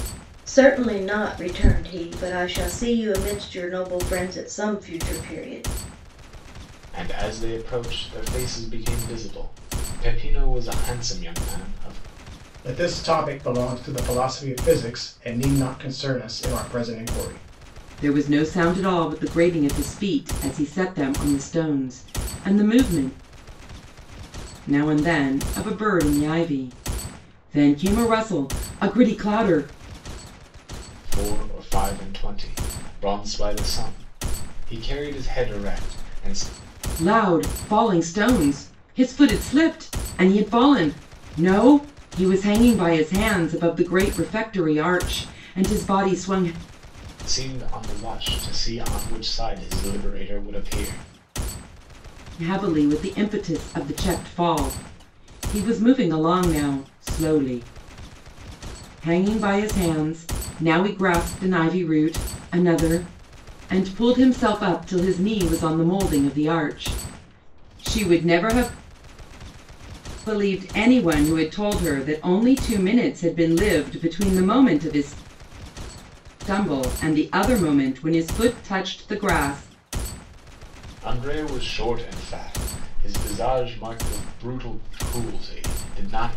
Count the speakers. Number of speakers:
4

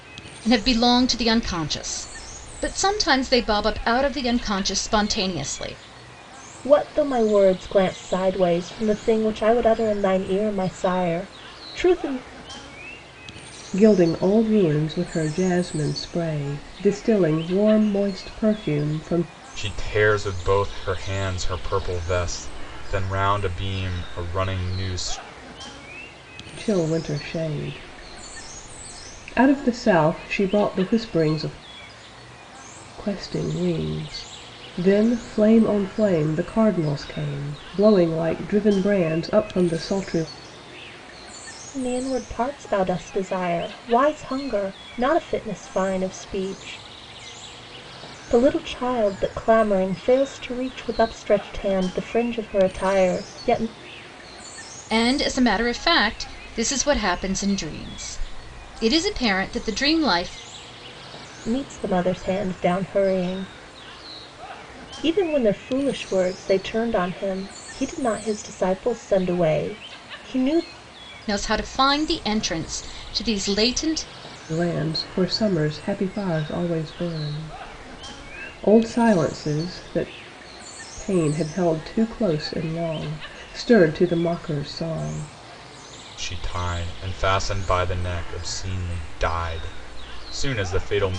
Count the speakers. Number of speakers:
4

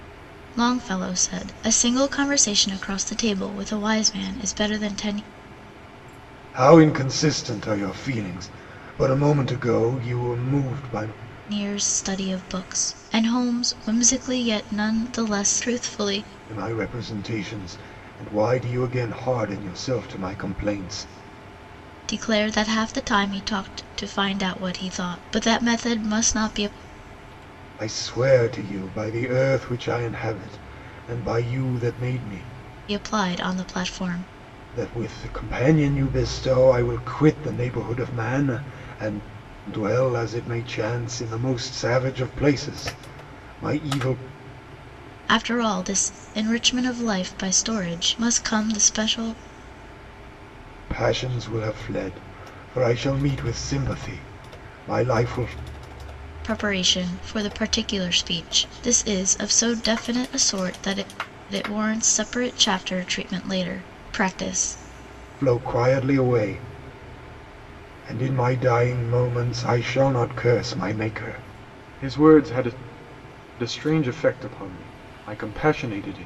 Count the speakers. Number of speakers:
2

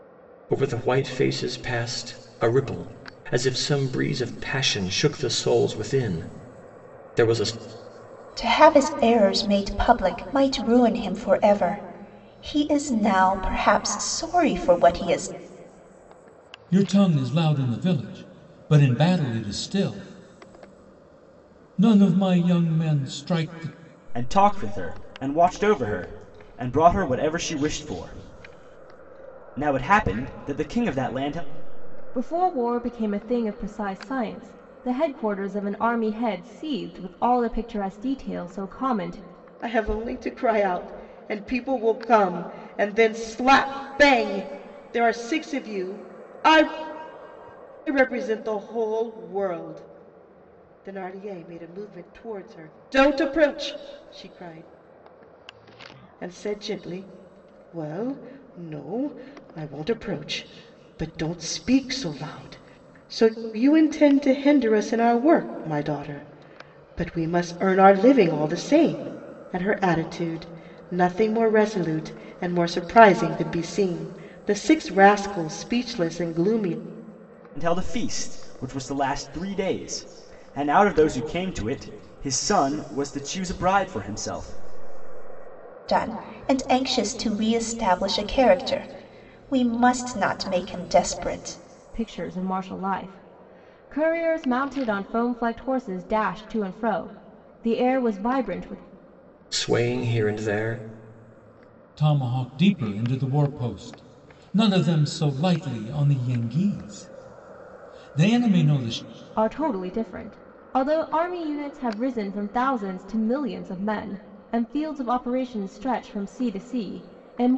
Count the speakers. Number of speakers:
6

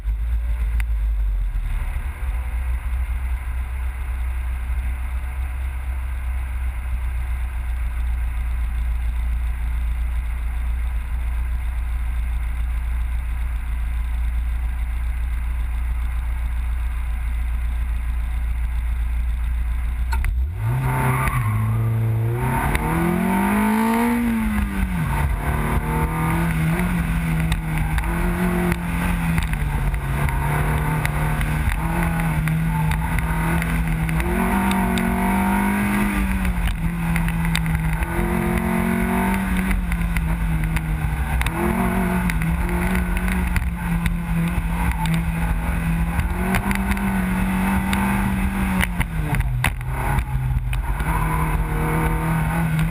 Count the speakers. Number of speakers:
0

